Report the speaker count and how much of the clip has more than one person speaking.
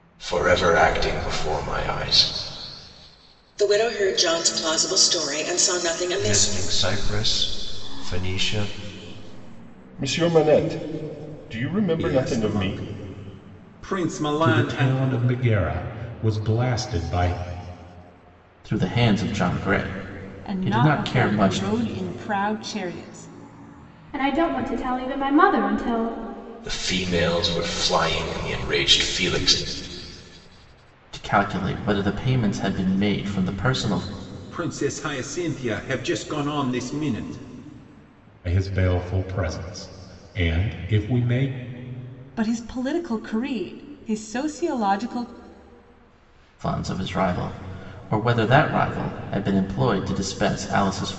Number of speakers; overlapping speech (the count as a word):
nine, about 6%